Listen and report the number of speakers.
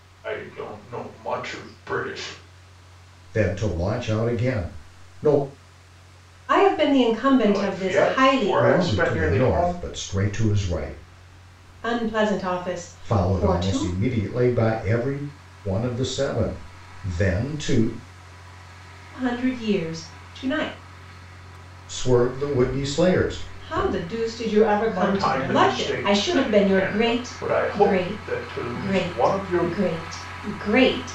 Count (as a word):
three